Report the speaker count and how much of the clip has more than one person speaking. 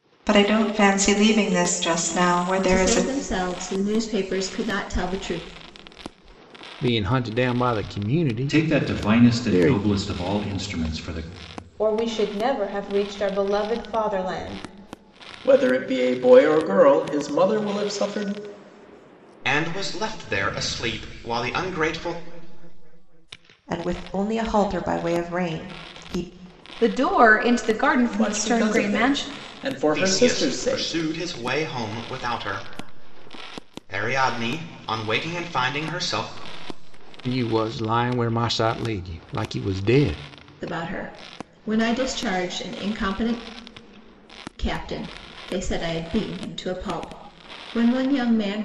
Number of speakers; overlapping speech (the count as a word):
nine, about 9%